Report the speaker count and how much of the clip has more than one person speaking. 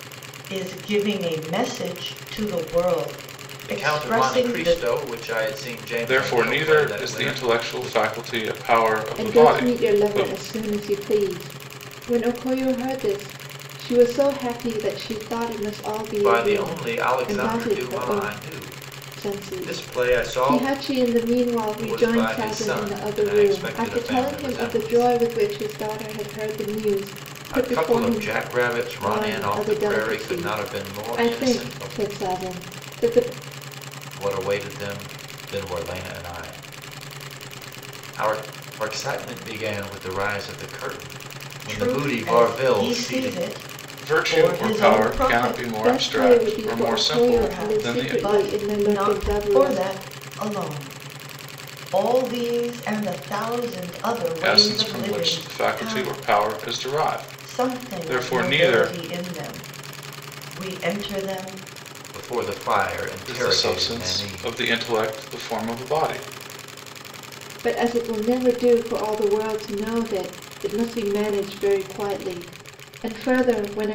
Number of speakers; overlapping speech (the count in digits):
4, about 37%